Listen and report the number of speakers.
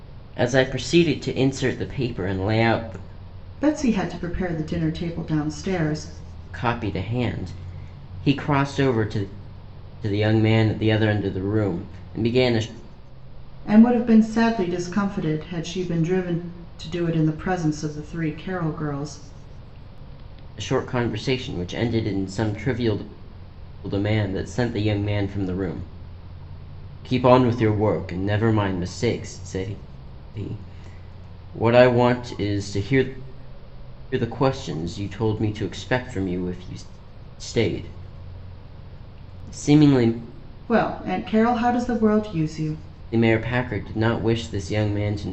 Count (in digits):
2